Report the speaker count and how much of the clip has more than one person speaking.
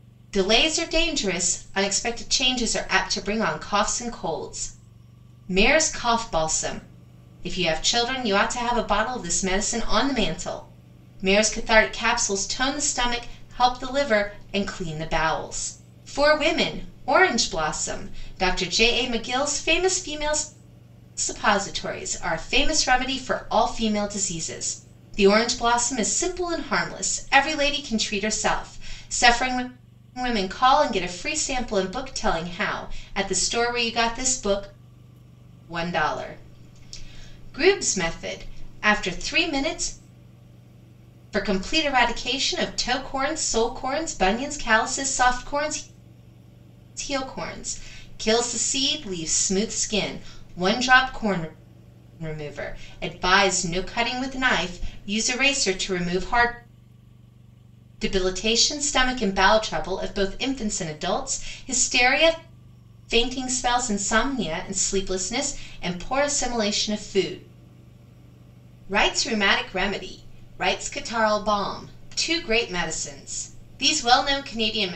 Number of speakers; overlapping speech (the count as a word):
one, no overlap